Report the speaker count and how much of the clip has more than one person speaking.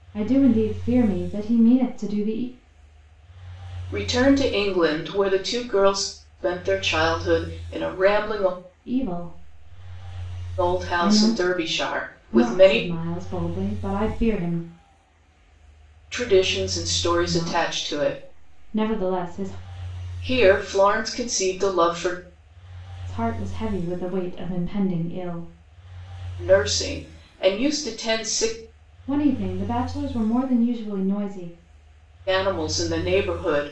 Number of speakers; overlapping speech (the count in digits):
2, about 7%